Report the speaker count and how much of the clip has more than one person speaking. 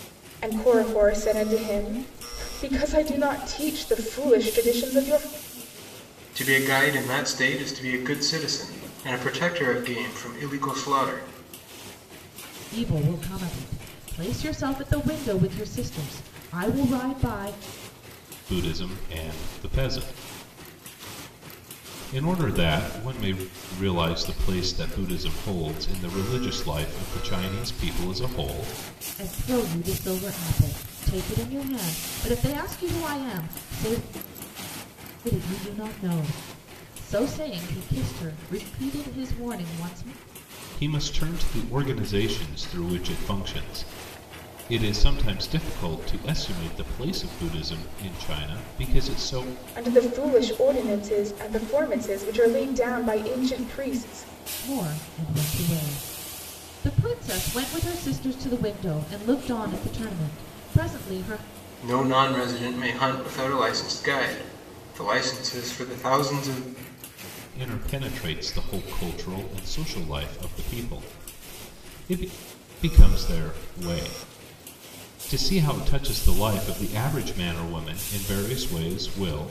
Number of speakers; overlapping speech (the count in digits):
4, no overlap